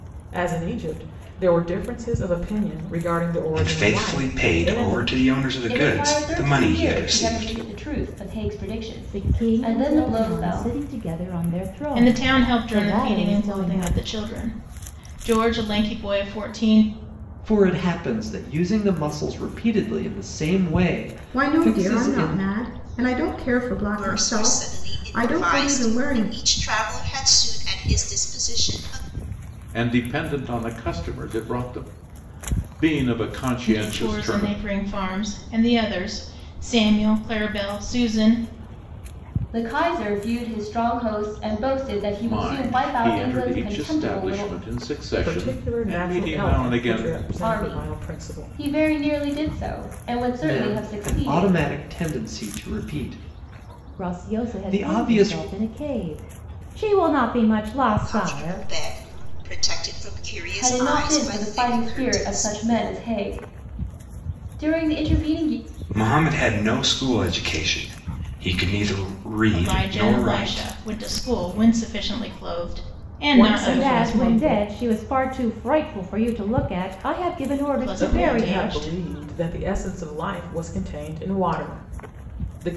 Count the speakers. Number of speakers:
9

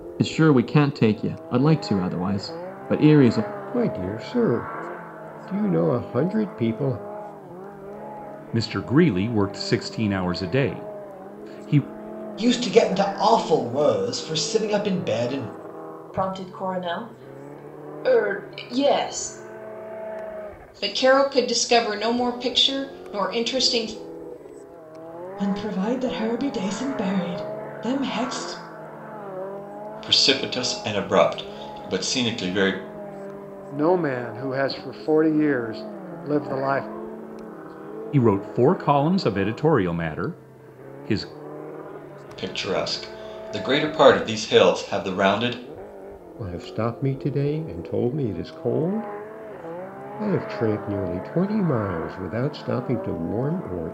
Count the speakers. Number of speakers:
9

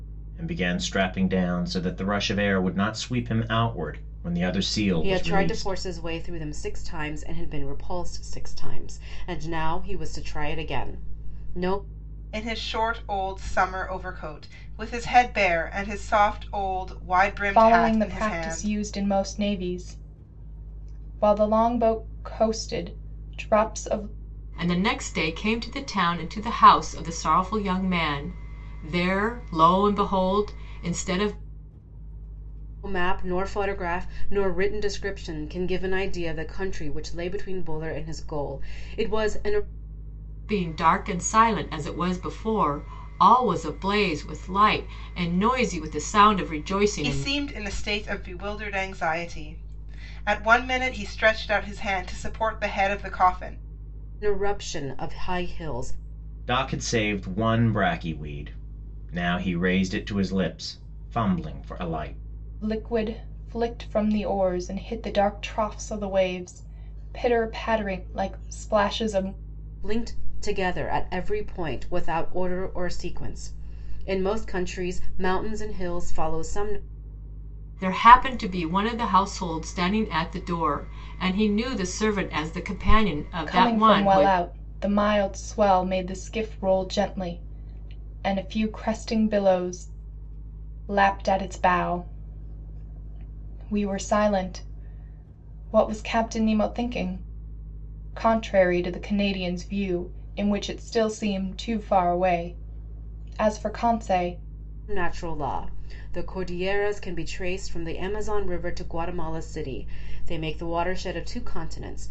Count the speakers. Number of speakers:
5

